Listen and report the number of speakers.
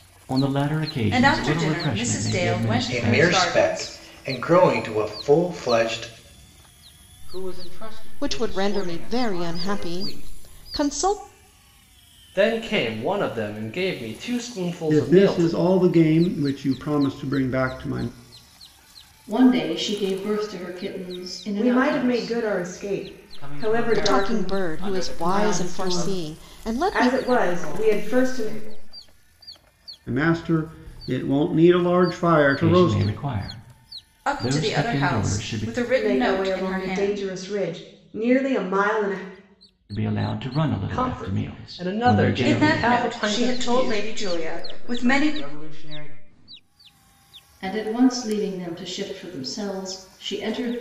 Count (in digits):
9